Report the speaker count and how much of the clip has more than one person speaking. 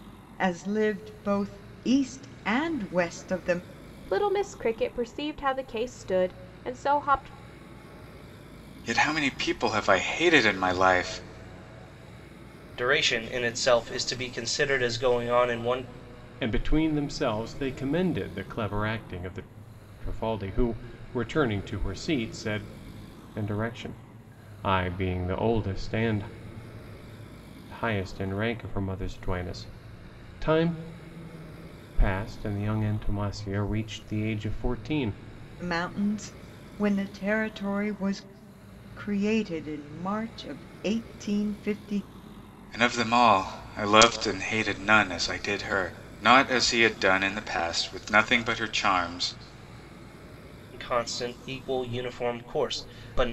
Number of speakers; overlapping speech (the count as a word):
five, no overlap